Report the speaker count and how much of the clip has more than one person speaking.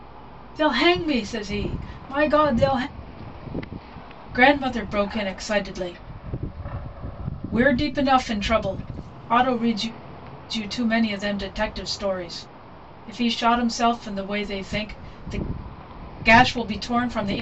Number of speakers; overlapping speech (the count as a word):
one, no overlap